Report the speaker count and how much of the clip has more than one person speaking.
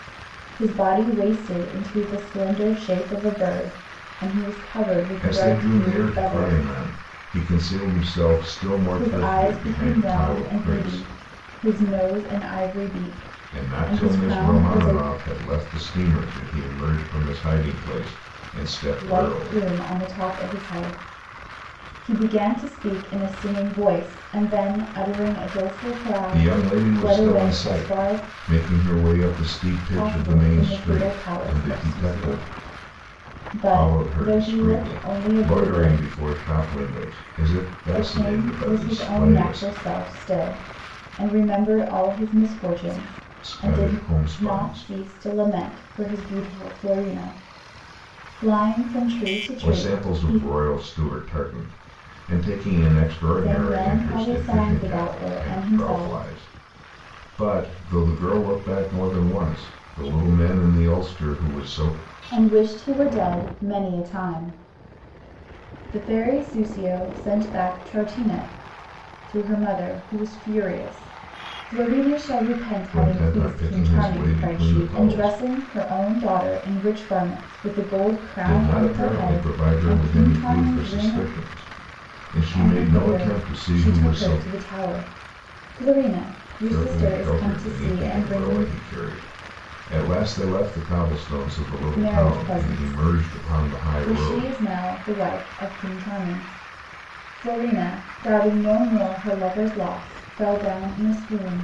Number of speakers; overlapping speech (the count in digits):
2, about 30%